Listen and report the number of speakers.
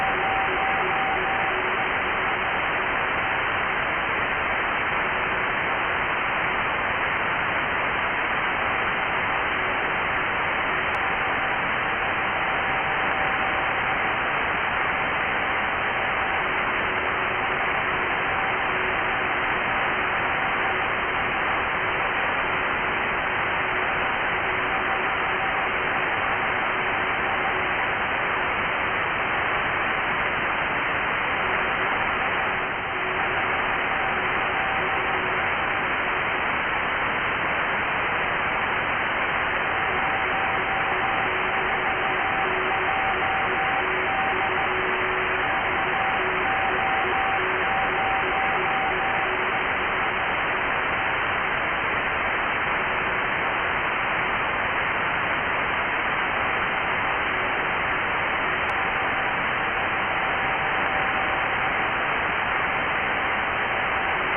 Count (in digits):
0